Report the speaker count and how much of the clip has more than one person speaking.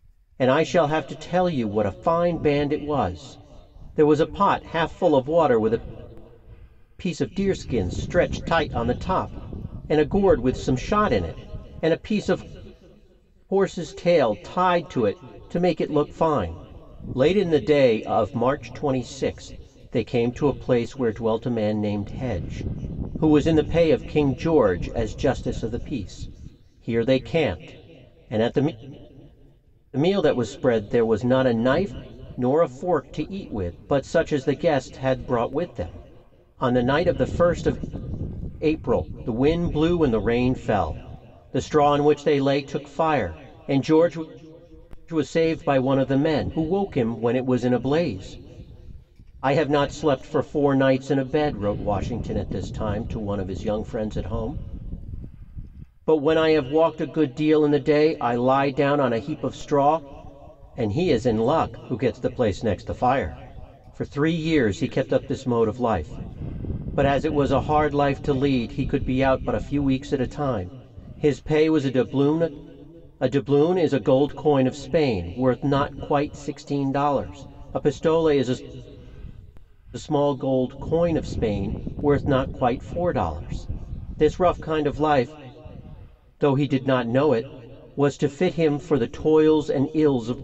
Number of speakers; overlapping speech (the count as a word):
one, no overlap